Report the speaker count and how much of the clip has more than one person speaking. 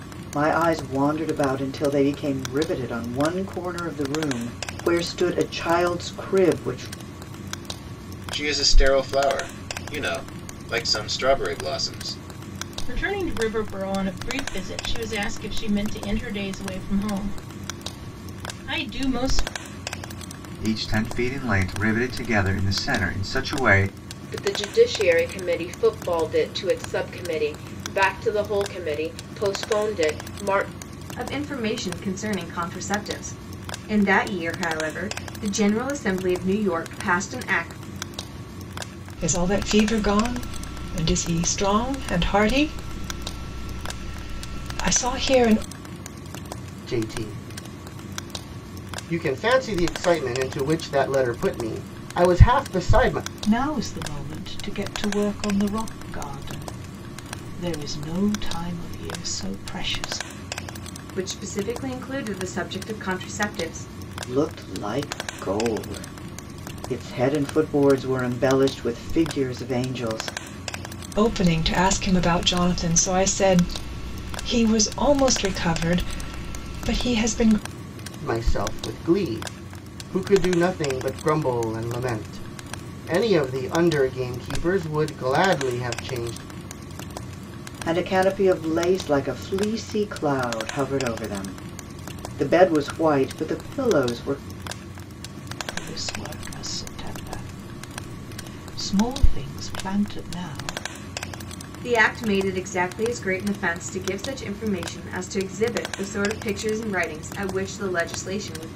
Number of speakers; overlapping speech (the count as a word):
nine, no overlap